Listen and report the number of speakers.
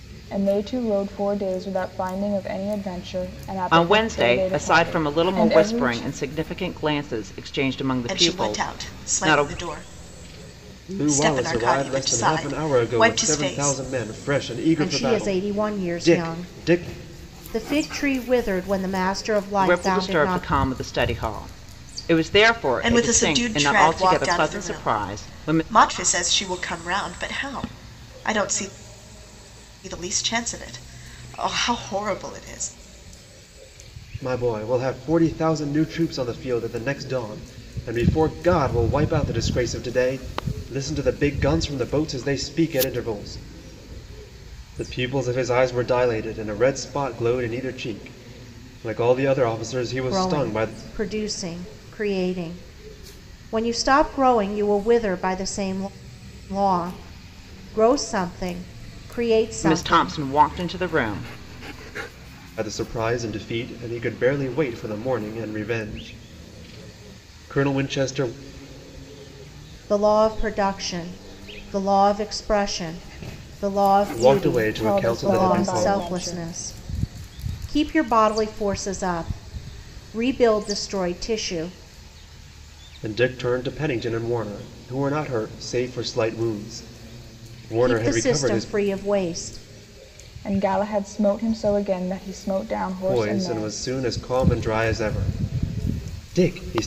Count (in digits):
5